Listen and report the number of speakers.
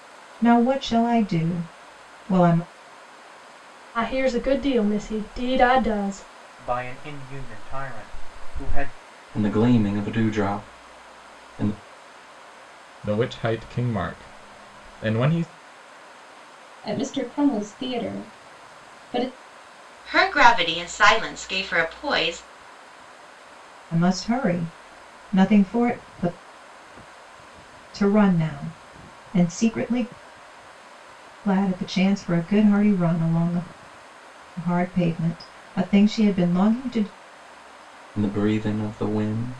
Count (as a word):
seven